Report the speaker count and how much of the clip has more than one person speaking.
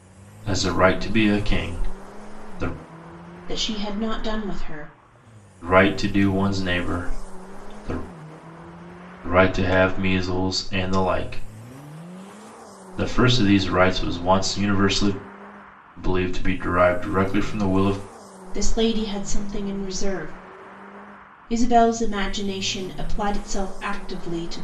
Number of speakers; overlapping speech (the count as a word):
two, no overlap